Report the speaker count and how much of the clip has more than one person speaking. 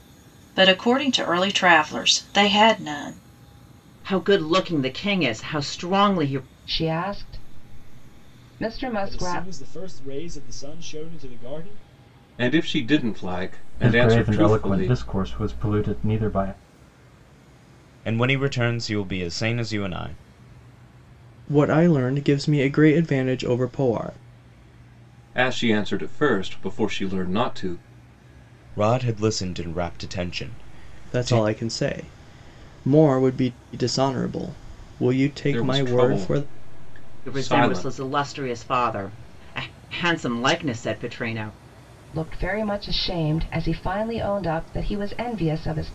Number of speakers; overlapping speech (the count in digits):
8, about 8%